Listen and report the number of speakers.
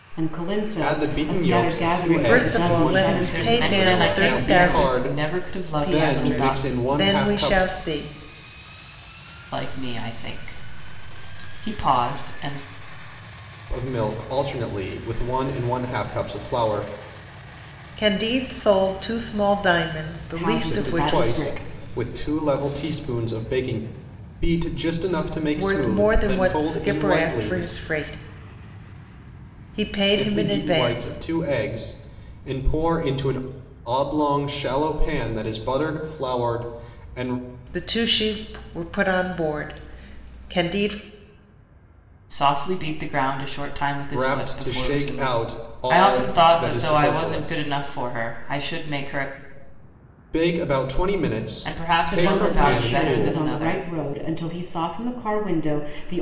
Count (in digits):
4